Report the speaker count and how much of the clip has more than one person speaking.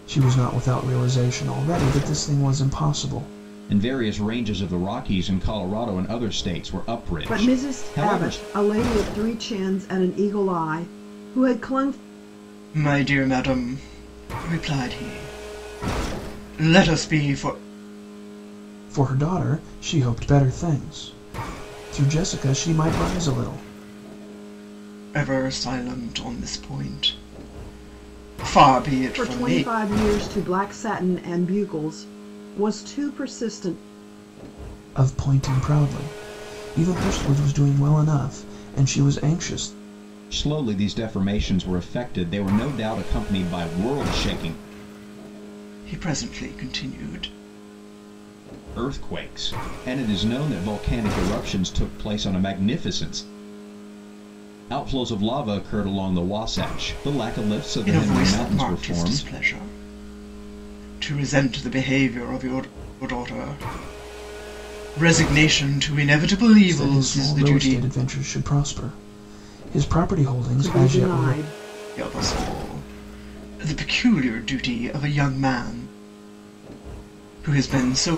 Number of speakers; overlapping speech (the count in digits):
4, about 7%